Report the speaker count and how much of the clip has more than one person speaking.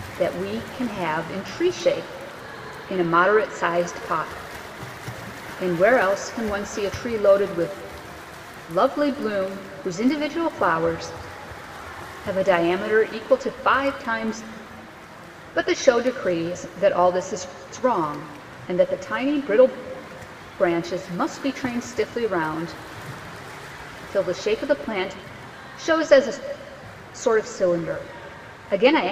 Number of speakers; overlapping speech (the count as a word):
one, no overlap